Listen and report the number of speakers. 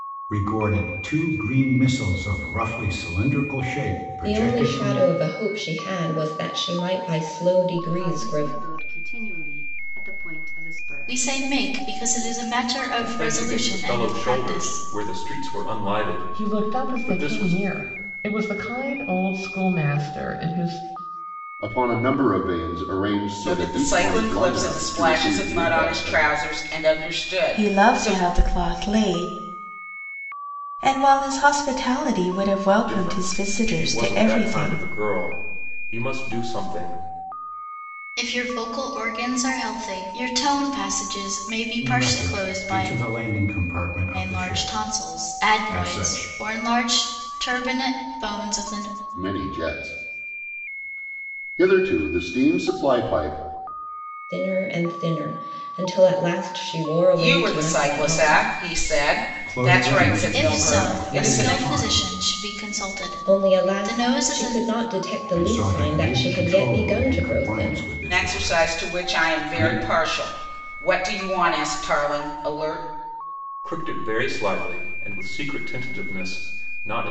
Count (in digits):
9